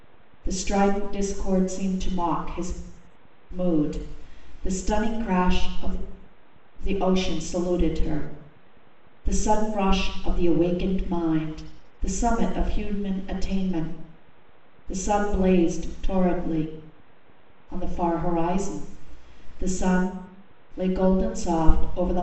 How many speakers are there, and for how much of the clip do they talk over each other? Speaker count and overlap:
1, no overlap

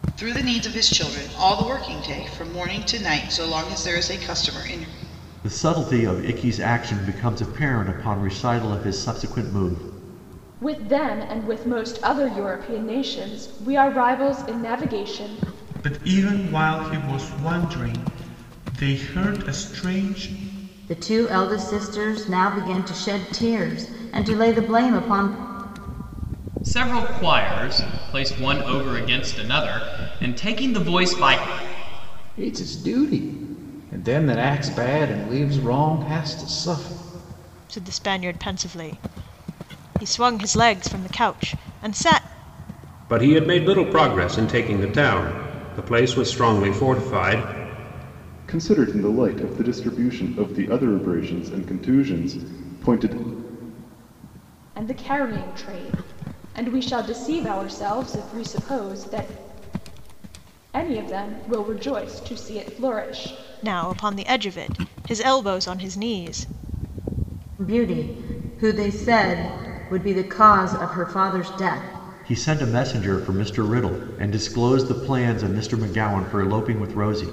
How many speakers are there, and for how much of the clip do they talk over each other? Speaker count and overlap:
10, no overlap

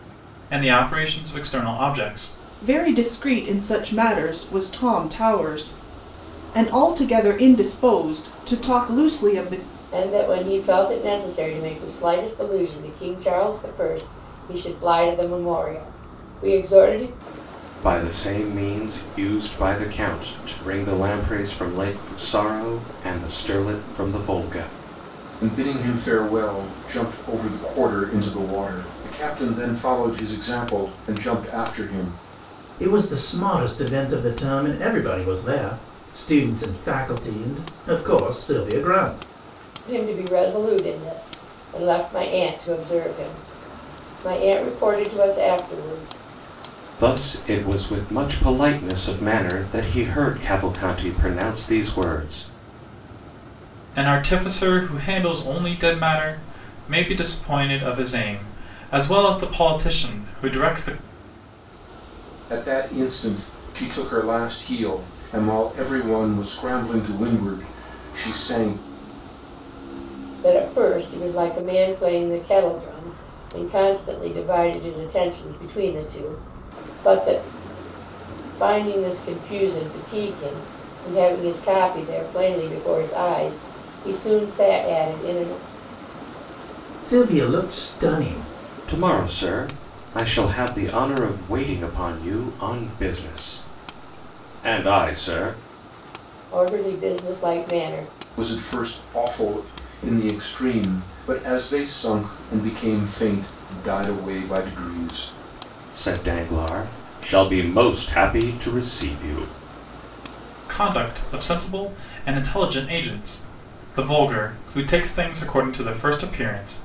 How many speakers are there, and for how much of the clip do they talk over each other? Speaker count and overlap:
6, no overlap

